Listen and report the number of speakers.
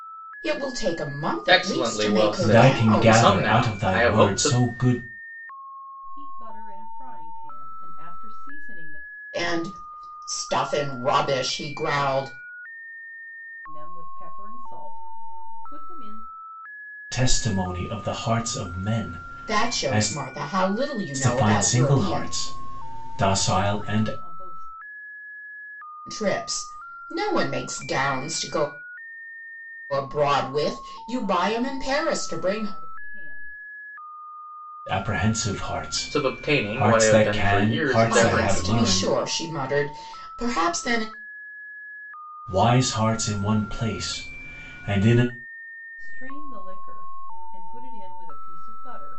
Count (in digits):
4